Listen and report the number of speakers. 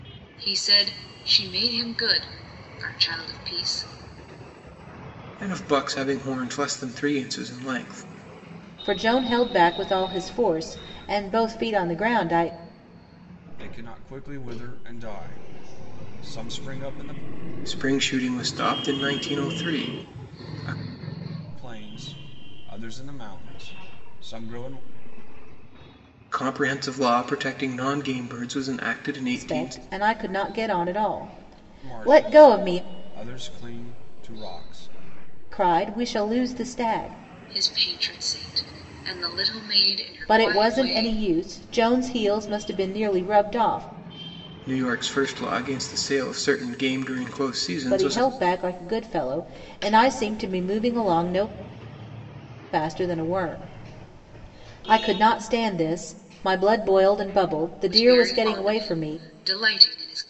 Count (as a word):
four